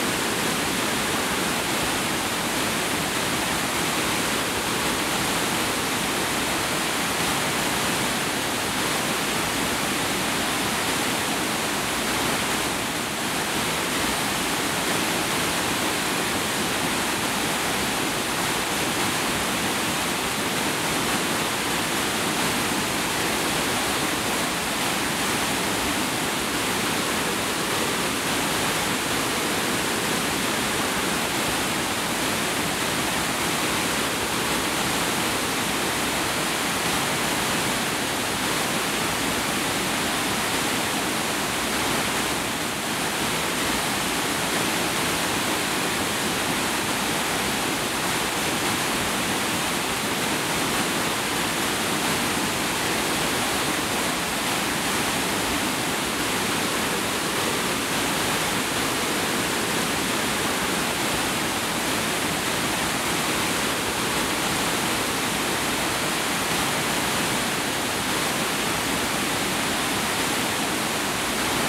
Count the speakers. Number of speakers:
0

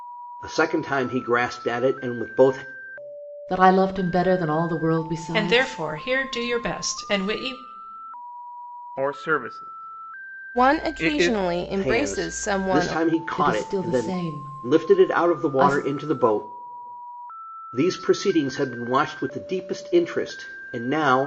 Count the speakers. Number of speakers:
5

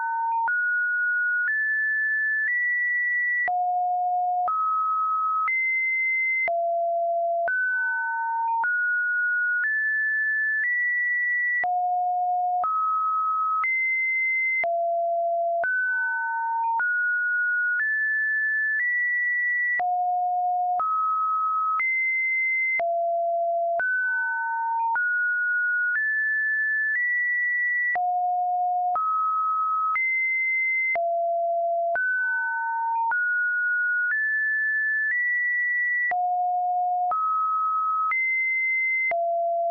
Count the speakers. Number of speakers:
0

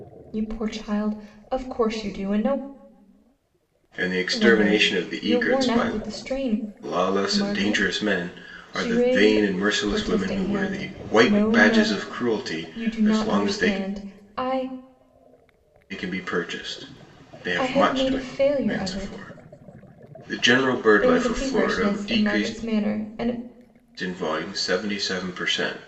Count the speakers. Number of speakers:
2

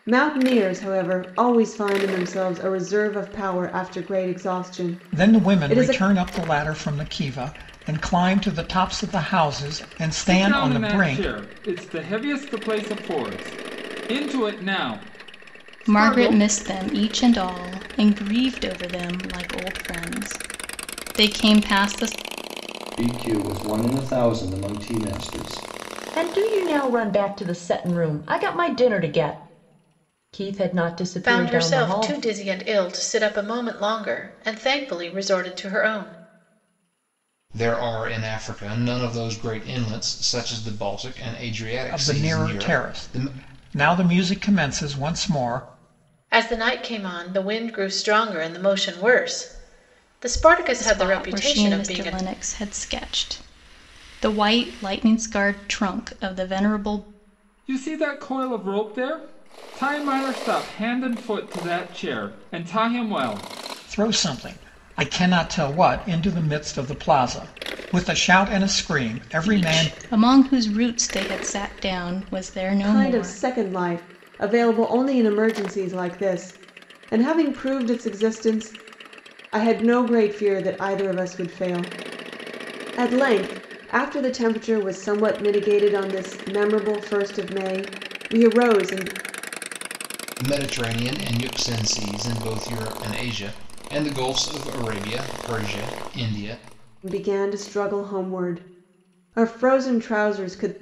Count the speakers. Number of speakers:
8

